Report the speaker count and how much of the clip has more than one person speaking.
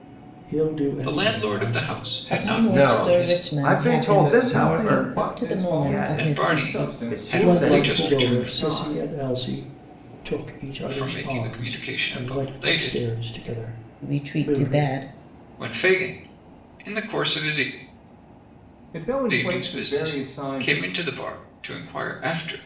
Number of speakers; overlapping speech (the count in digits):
5, about 56%